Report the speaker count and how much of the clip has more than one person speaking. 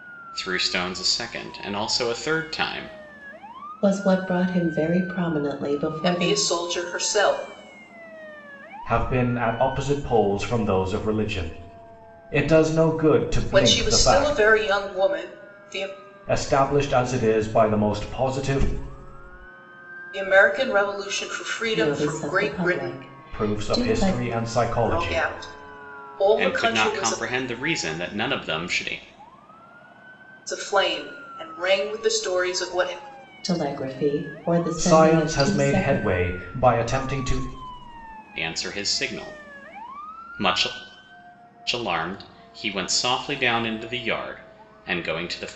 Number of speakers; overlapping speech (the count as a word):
four, about 14%